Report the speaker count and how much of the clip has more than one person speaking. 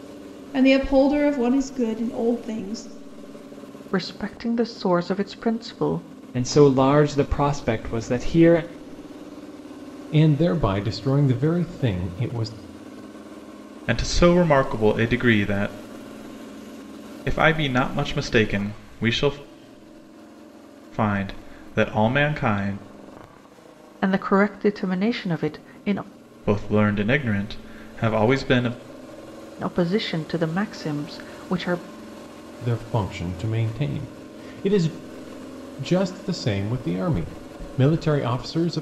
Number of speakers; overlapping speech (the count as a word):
five, no overlap